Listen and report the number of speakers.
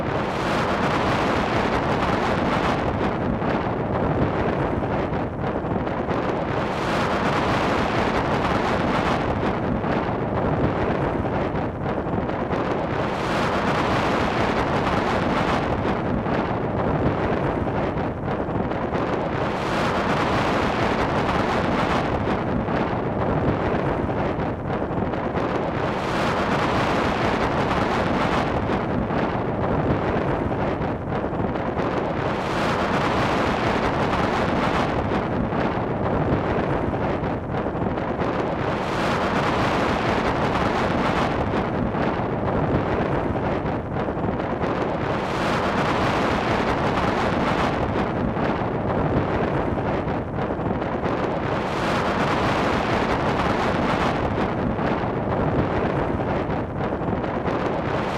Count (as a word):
zero